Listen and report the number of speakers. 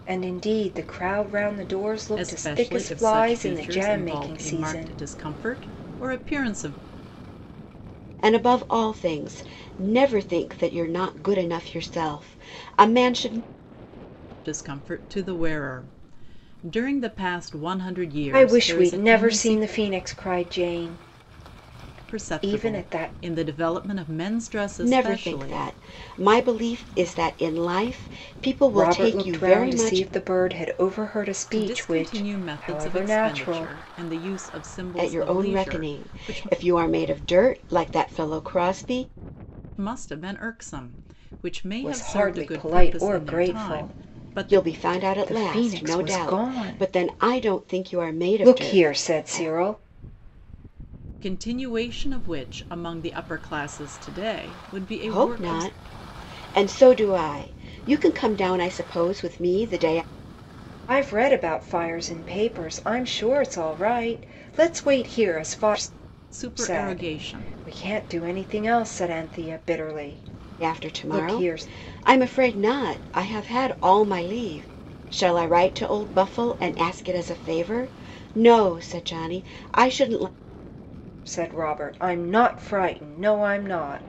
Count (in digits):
3